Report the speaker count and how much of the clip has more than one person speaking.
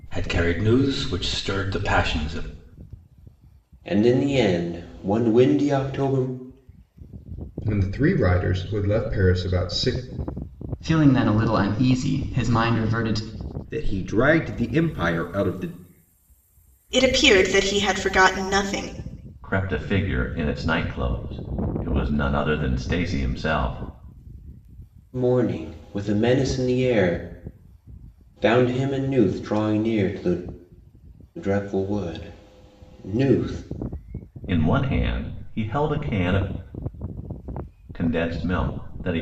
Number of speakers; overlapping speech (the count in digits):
7, no overlap